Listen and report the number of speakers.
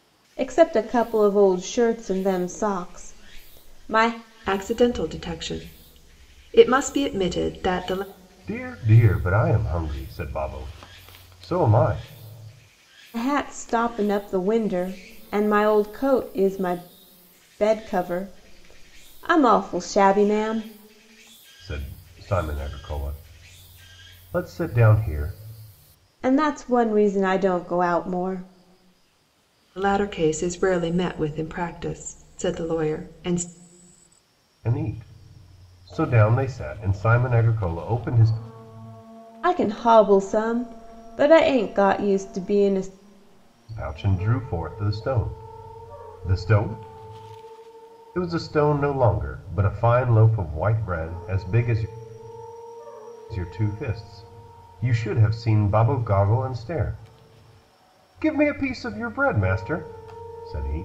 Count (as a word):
three